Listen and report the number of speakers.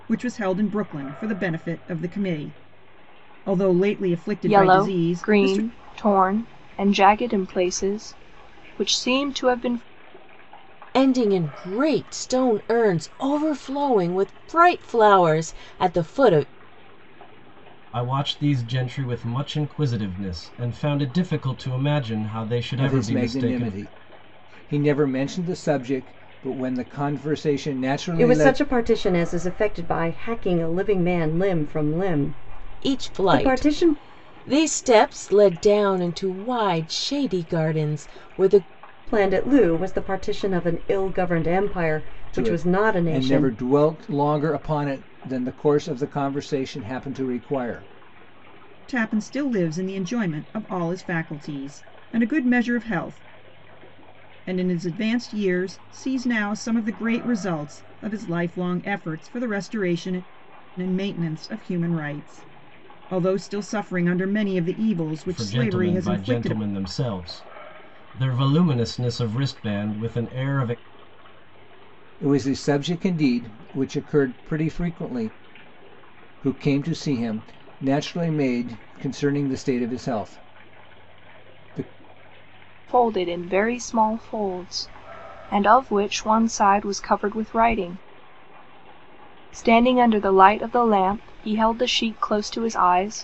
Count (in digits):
6